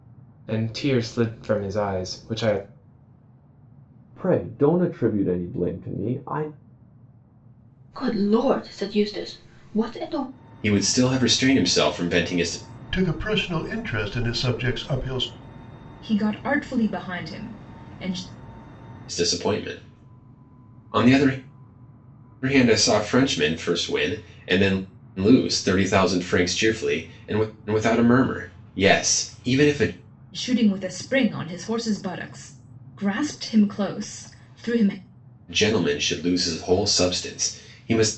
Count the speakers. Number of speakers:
six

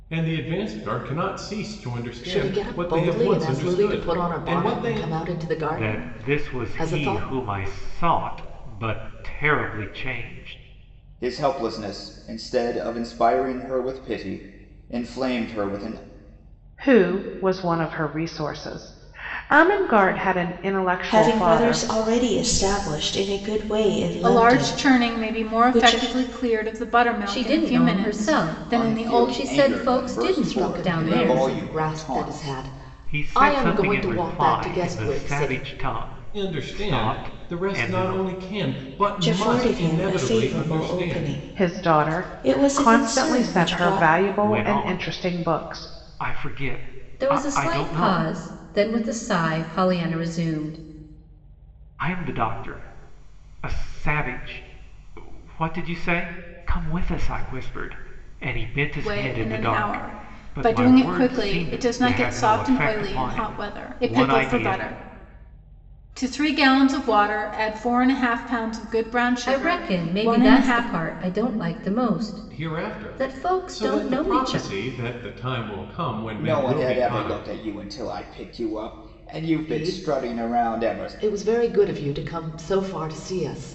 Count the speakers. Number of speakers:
eight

